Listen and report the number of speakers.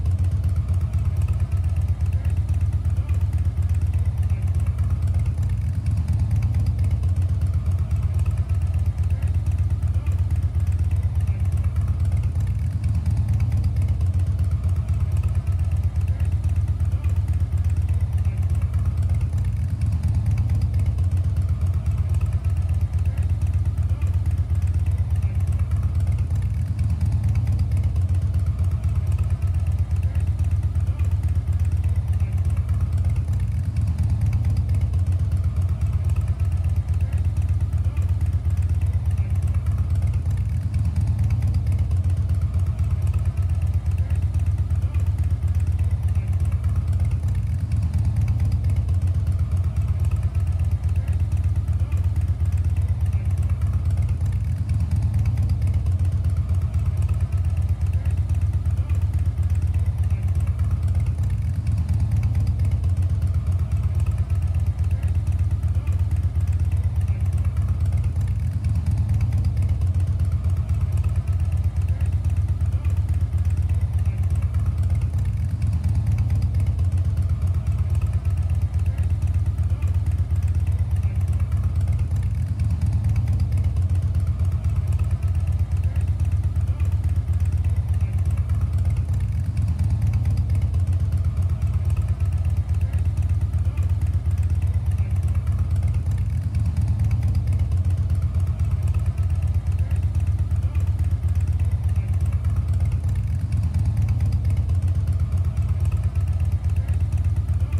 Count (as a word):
zero